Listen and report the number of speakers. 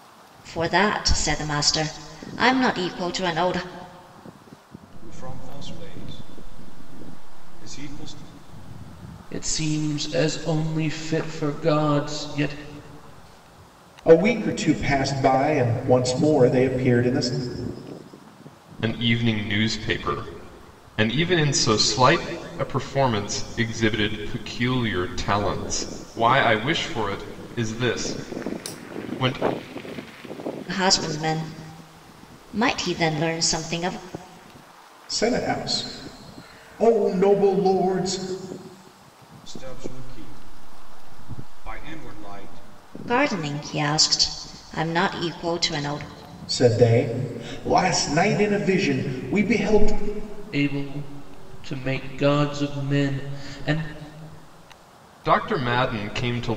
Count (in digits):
5